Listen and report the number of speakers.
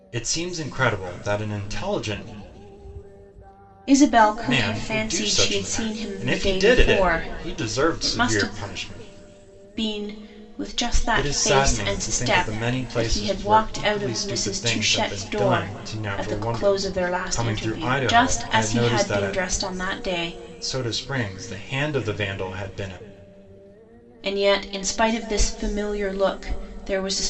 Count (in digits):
2